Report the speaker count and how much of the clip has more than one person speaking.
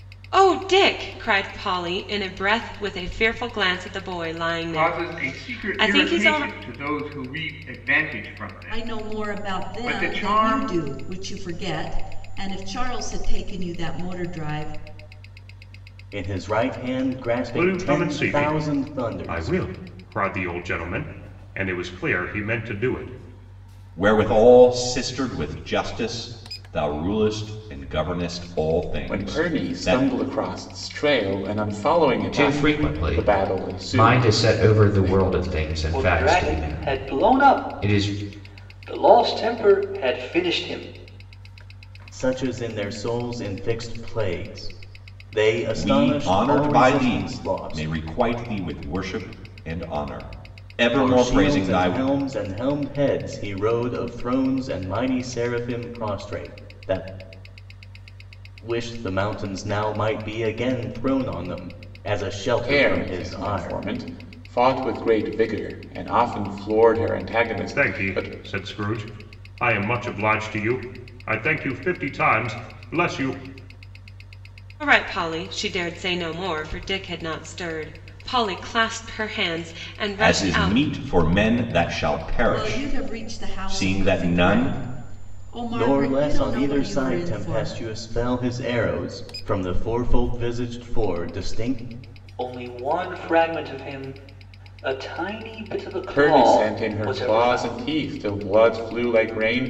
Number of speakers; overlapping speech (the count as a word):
nine, about 24%